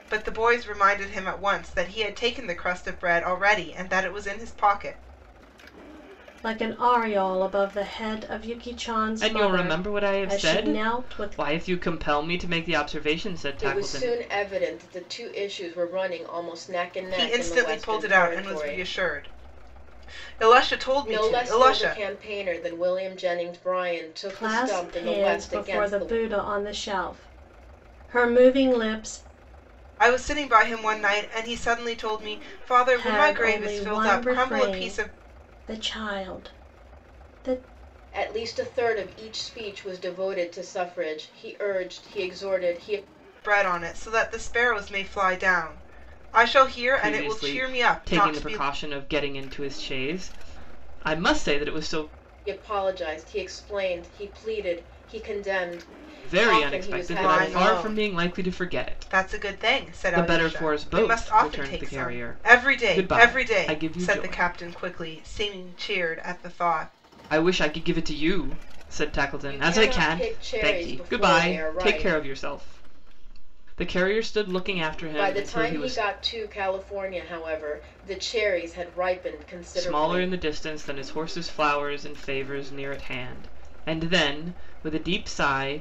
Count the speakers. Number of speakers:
four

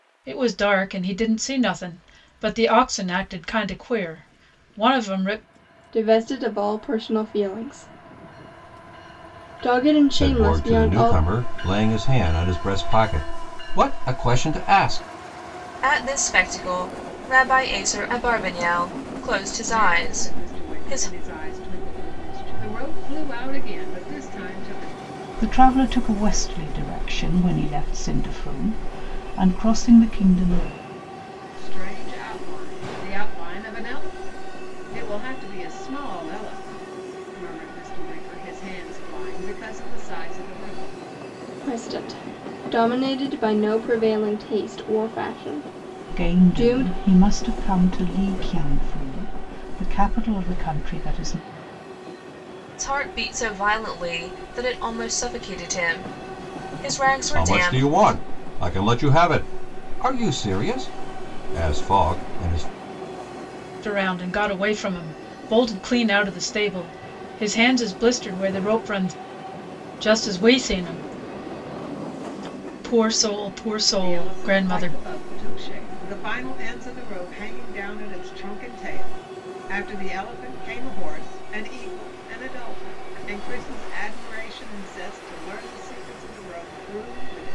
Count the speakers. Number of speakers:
six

